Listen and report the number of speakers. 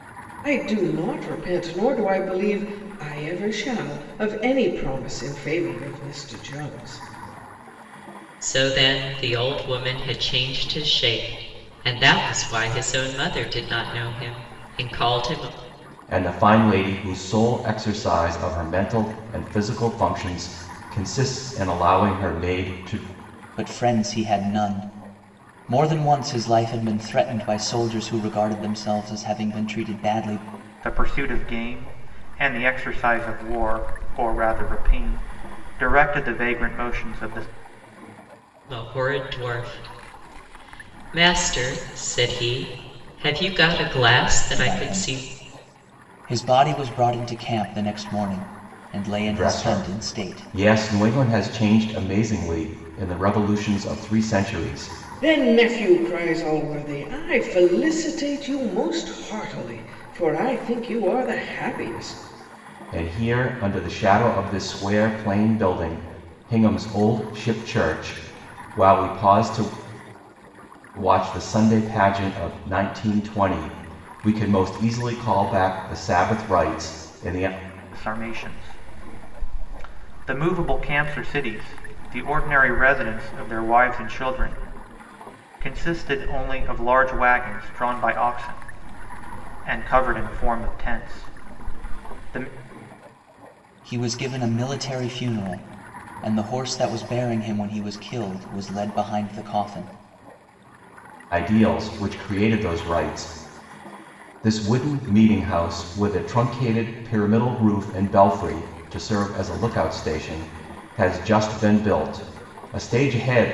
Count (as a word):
five